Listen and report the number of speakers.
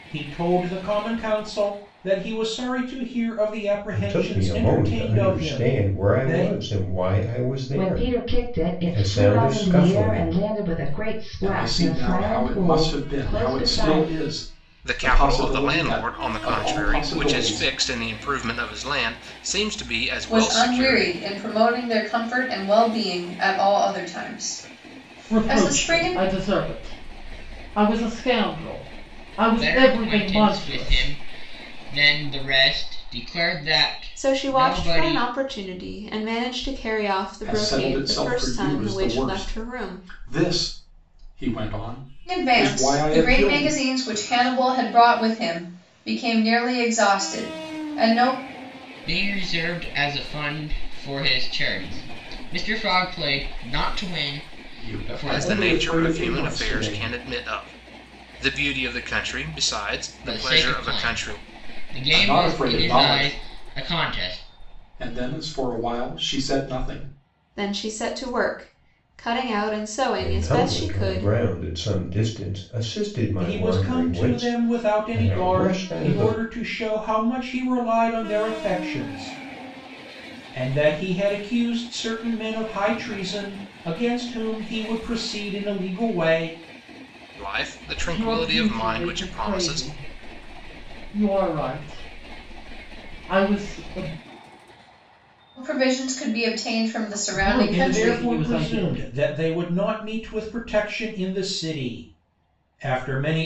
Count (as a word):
nine